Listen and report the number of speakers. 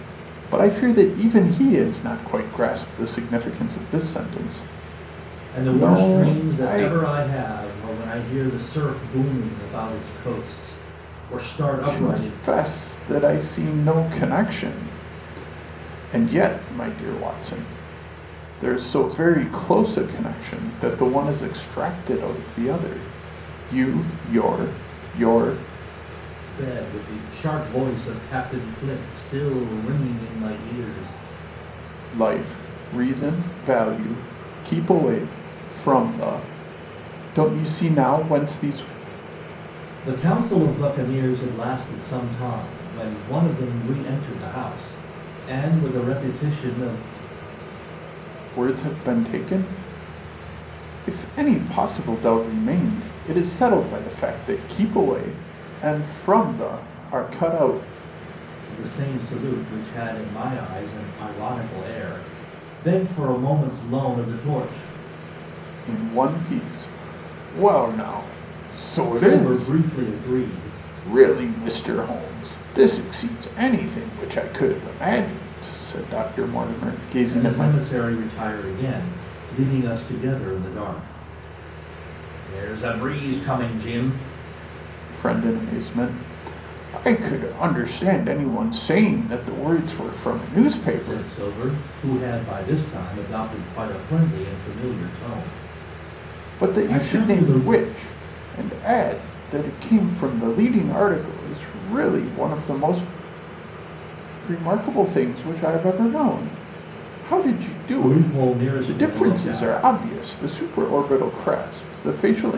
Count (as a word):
two